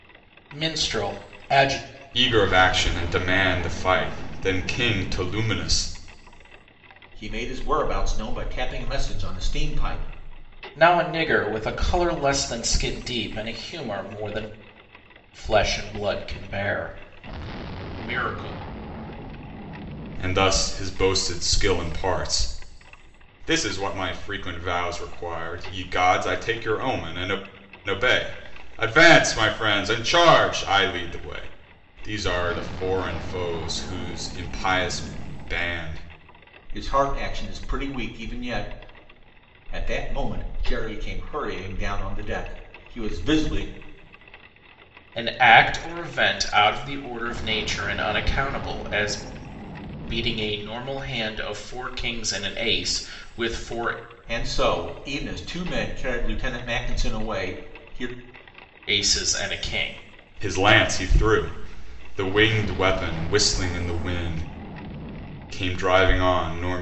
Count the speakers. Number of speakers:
3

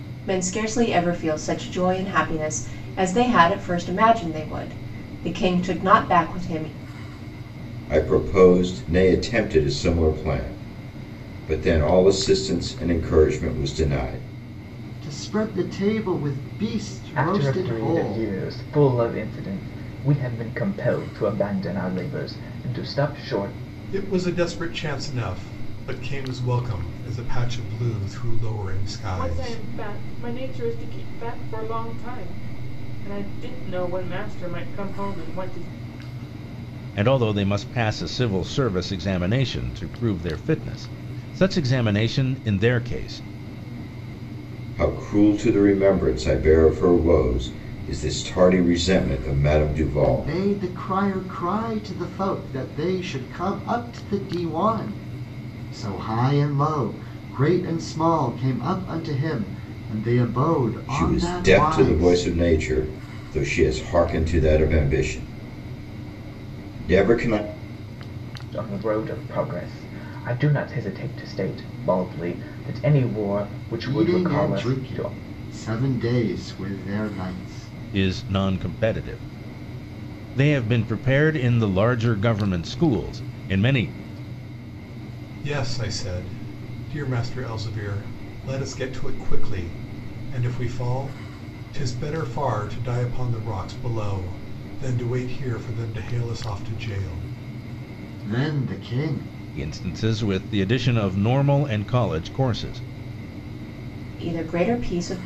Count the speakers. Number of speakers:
7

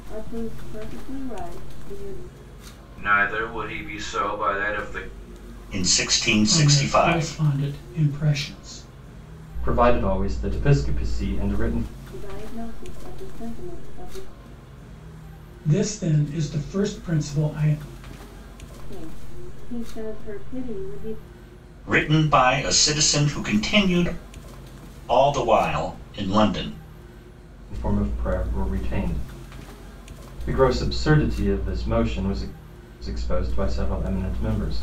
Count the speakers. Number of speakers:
5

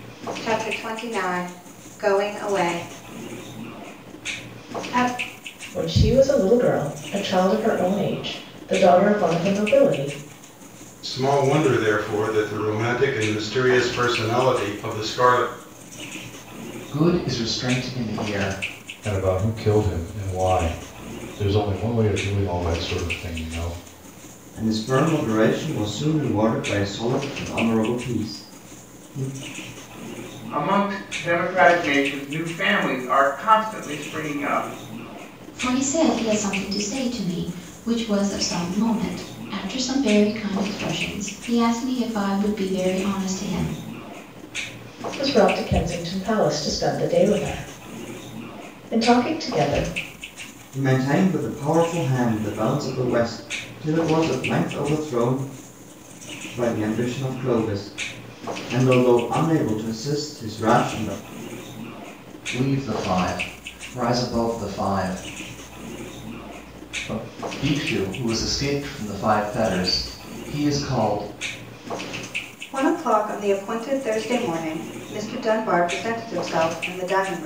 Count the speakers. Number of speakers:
8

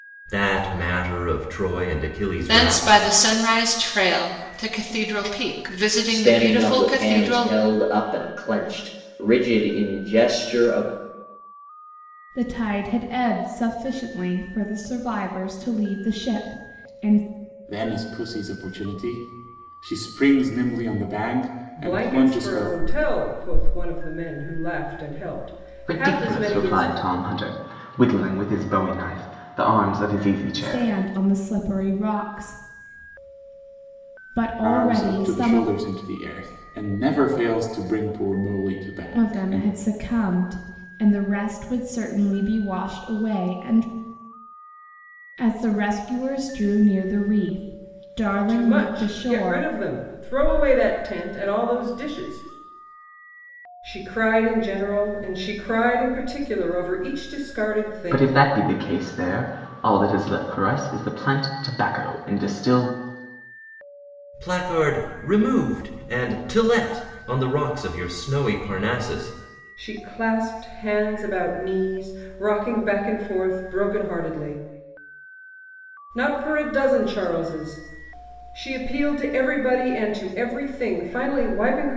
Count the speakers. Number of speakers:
7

